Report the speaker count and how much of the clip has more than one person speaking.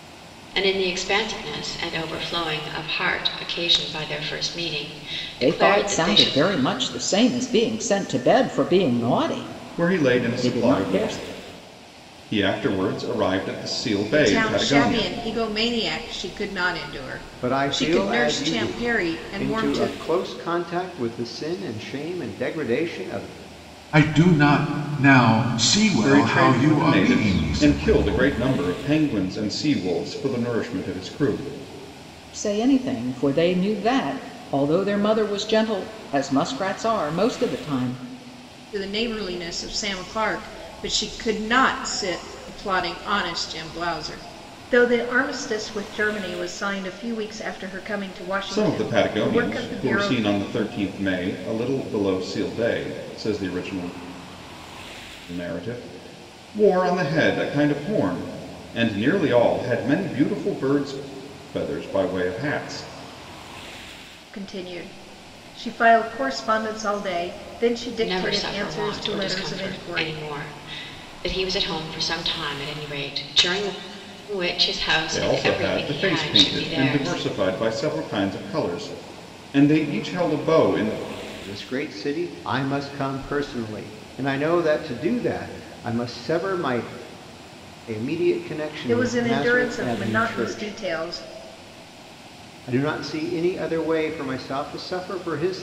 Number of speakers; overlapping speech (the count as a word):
six, about 17%